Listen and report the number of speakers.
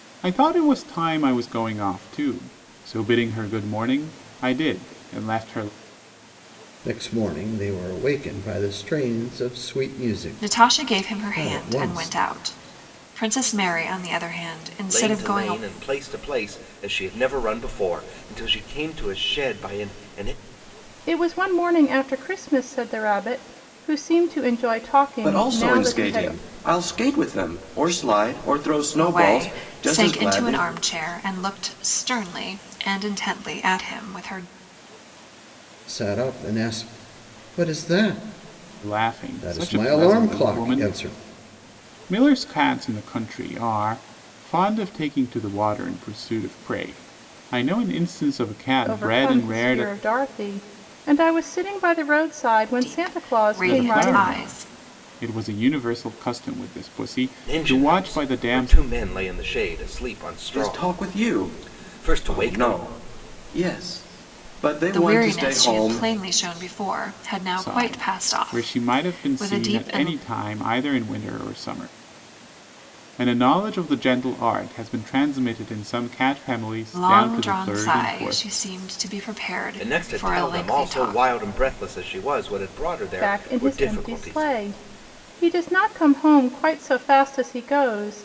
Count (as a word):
six